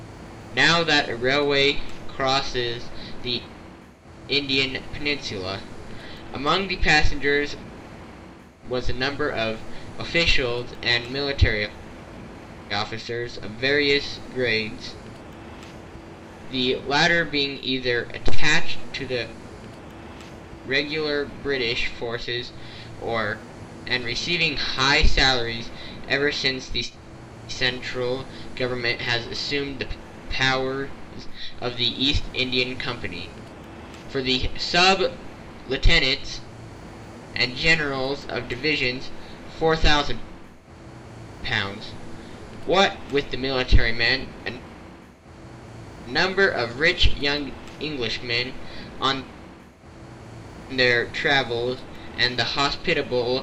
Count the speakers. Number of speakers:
one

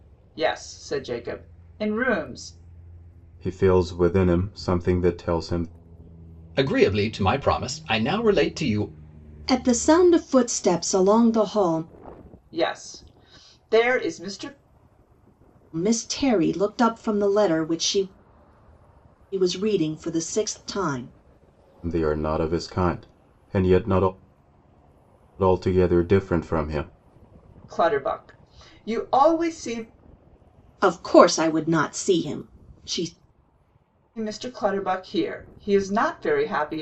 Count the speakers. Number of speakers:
four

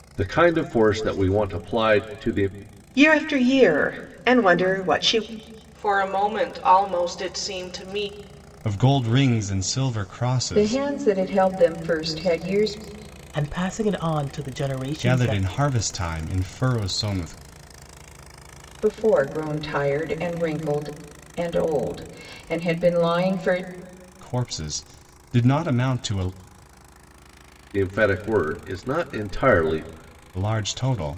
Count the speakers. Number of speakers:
six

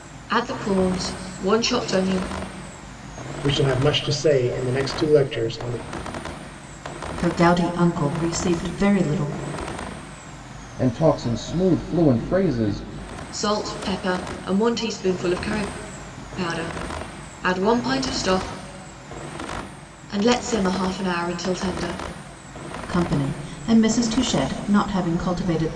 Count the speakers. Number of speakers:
four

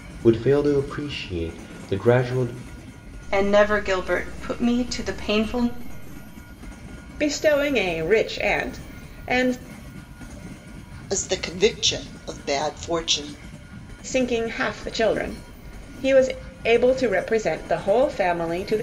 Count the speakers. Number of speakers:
four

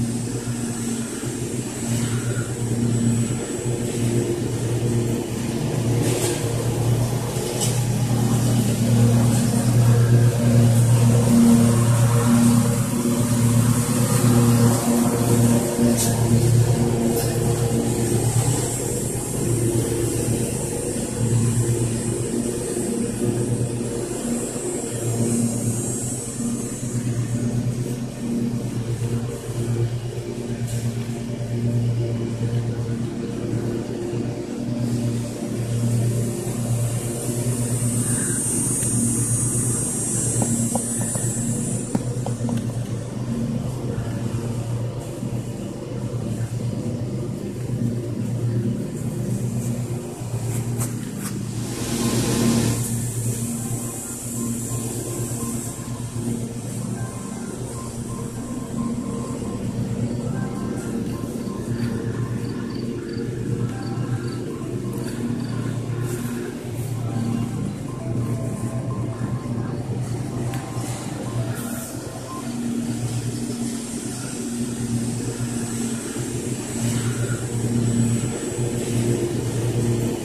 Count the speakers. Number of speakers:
zero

